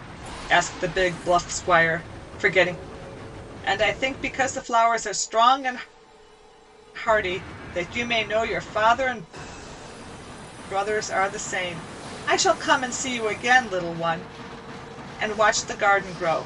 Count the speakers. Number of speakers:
one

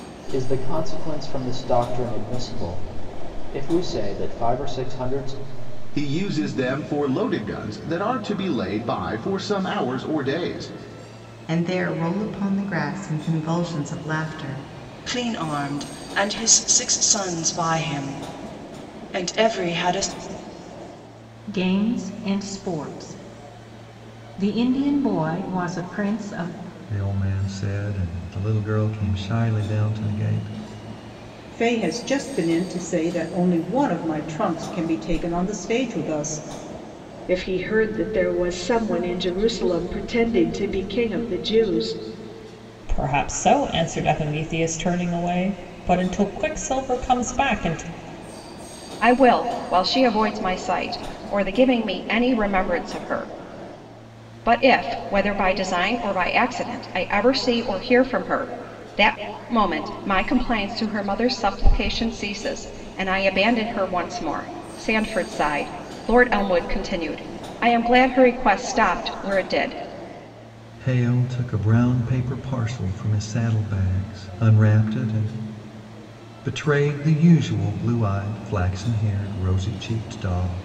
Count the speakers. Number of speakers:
ten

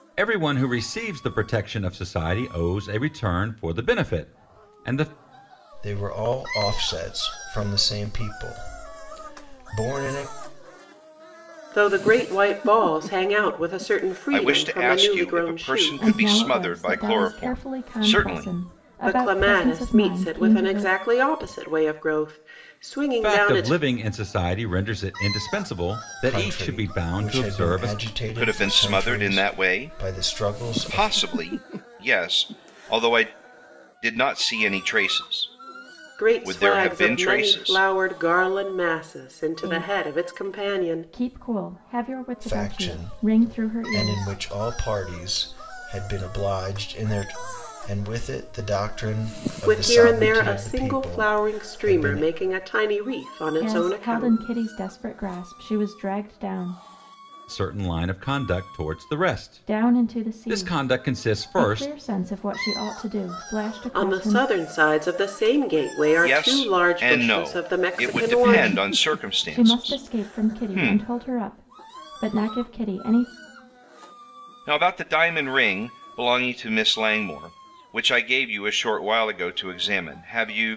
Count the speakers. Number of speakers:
five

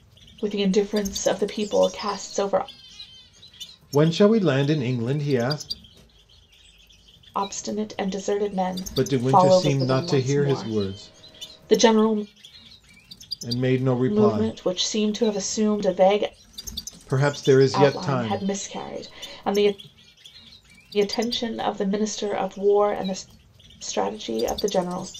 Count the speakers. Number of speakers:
two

